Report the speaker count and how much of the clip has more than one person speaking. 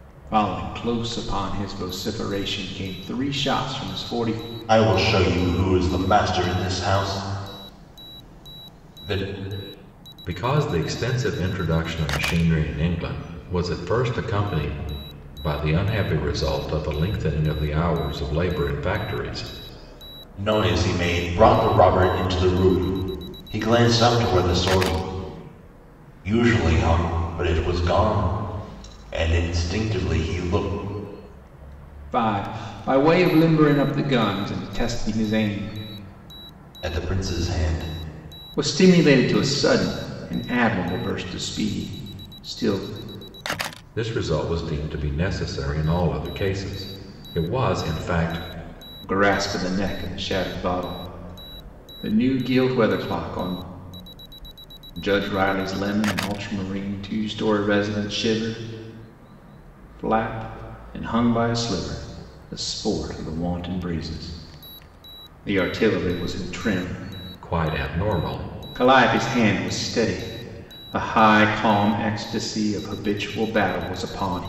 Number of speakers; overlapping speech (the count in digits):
3, no overlap